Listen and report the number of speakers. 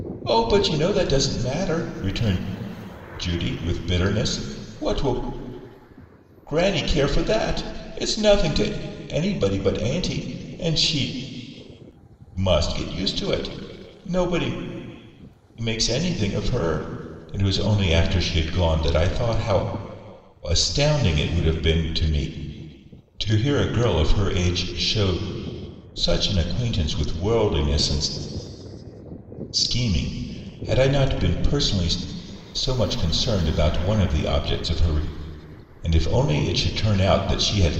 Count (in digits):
1